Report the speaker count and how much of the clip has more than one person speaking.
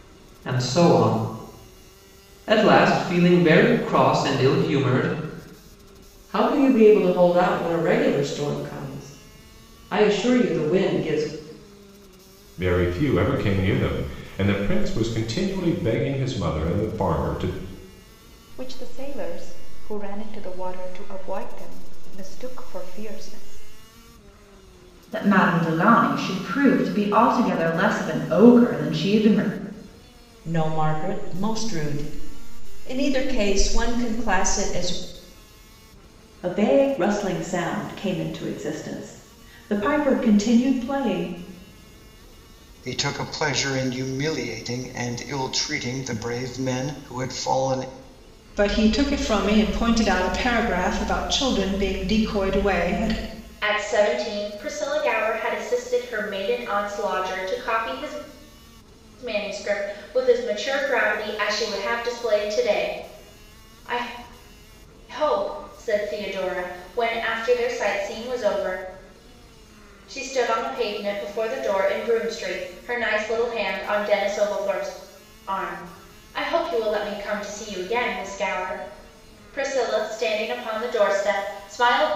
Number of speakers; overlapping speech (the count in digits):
10, no overlap